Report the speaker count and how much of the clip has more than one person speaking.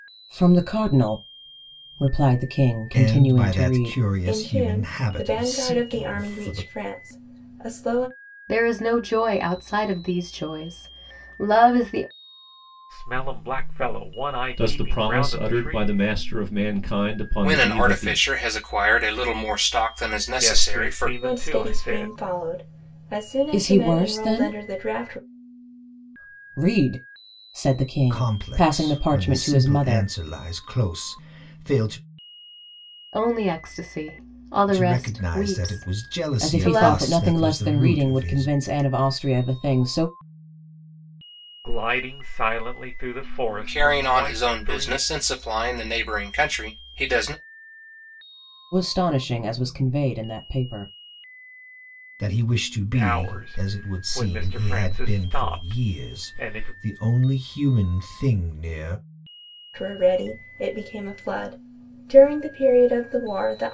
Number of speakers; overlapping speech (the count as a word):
seven, about 32%